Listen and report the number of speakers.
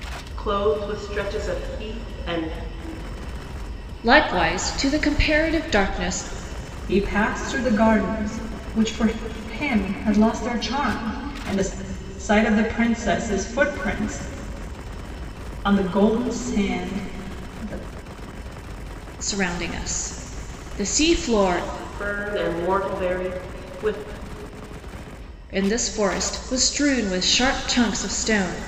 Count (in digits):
3